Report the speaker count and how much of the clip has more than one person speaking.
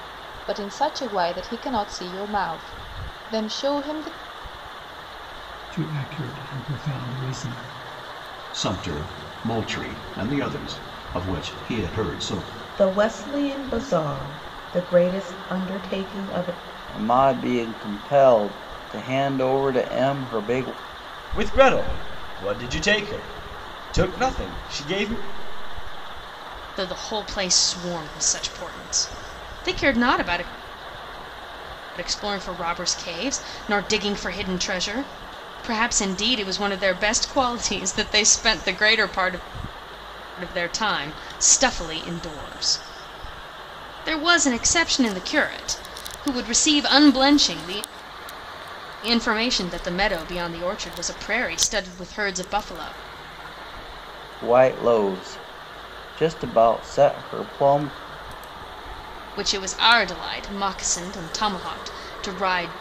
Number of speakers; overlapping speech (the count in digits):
7, no overlap